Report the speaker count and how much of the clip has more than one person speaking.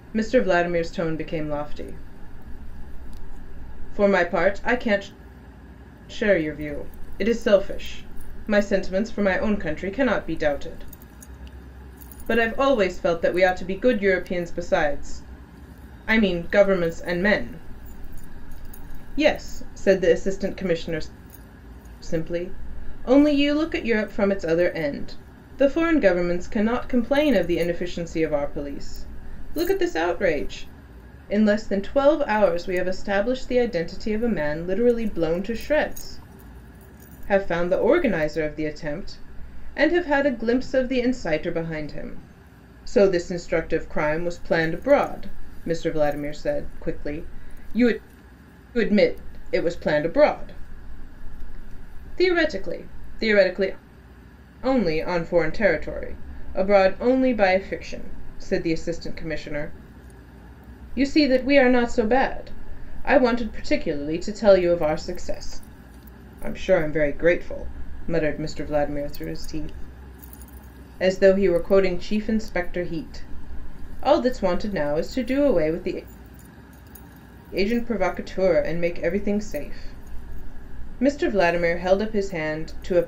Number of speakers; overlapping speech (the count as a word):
one, no overlap